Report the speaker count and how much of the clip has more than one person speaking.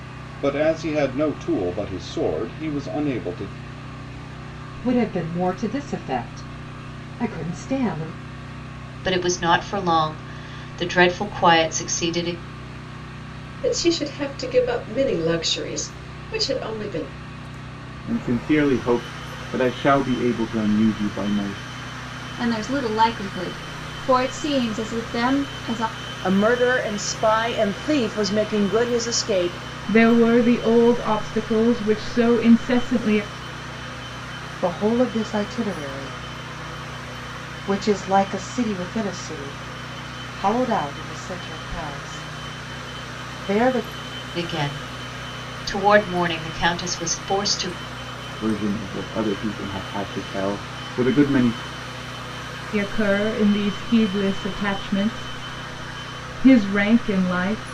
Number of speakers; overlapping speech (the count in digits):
9, no overlap